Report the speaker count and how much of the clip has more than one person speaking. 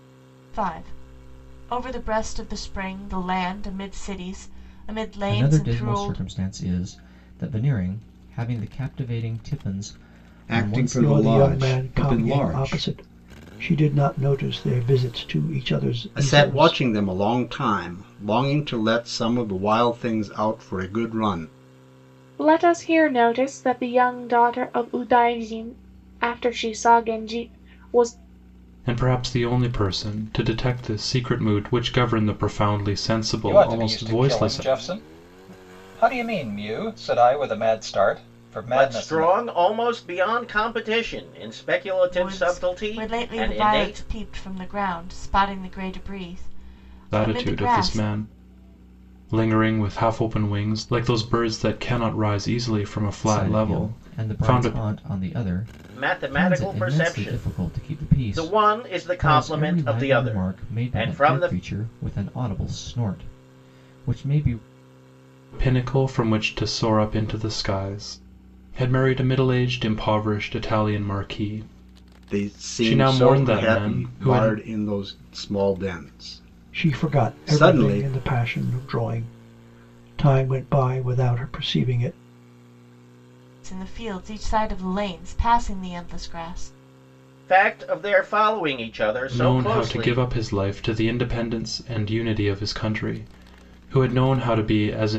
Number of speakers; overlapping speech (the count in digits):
9, about 21%